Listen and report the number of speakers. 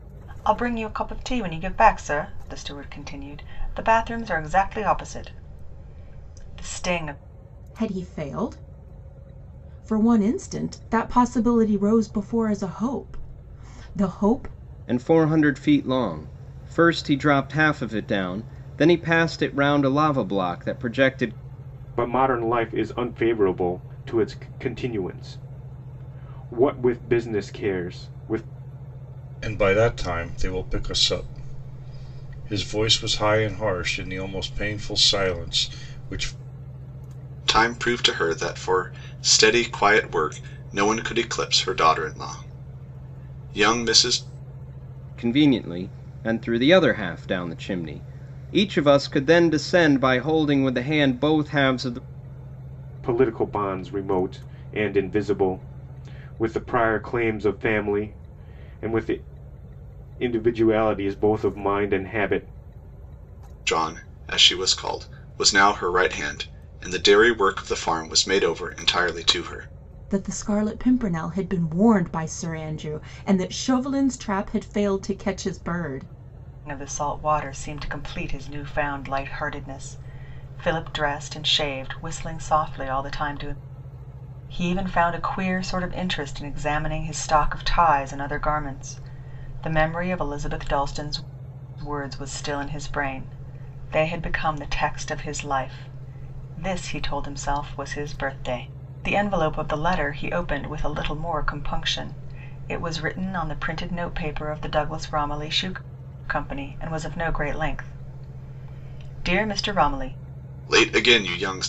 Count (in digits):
6